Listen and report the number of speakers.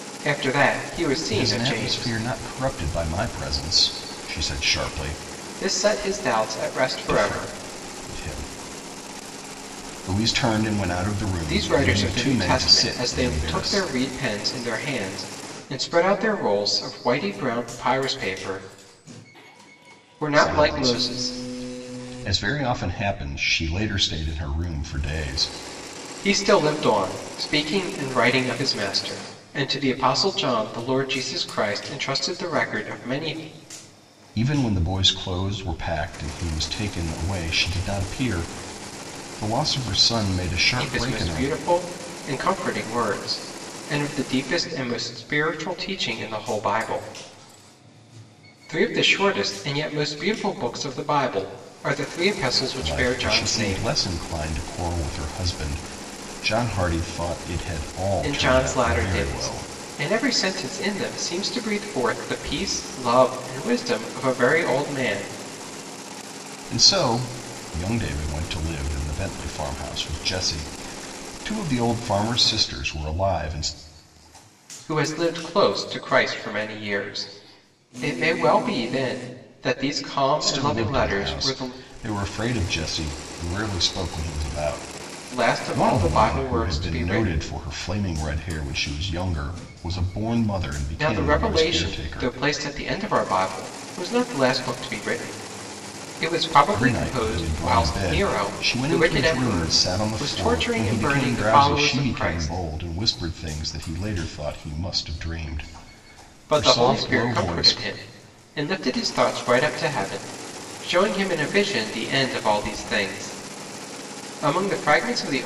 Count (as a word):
two